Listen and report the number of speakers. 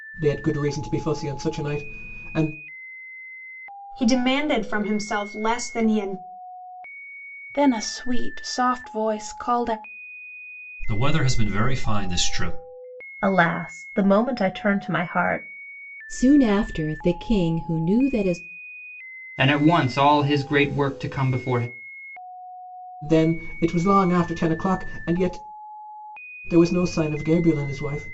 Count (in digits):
7